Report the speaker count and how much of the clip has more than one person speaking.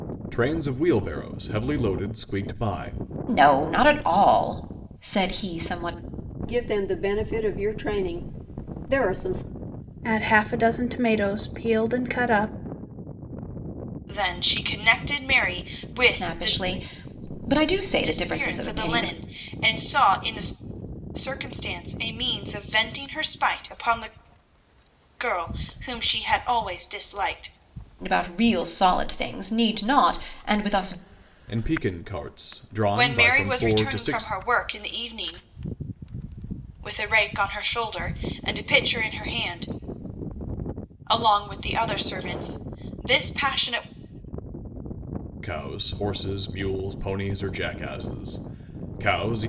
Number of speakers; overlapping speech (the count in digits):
5, about 6%